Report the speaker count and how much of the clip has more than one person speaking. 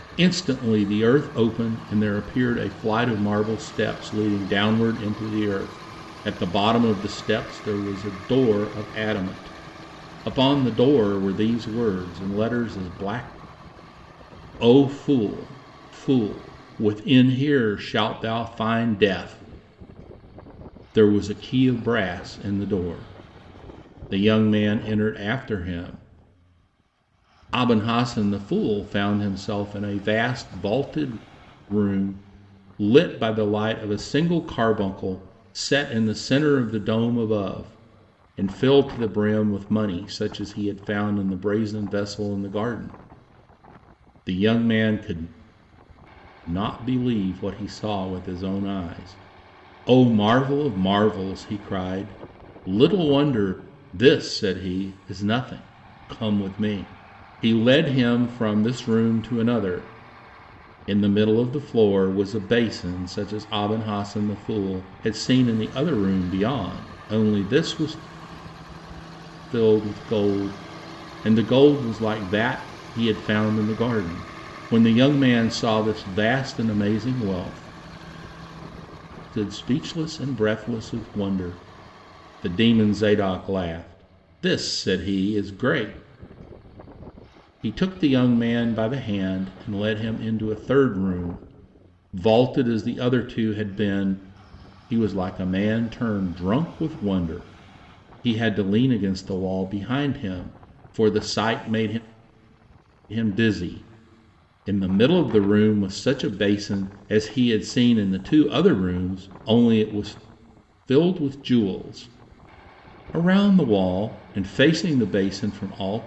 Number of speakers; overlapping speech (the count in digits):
1, no overlap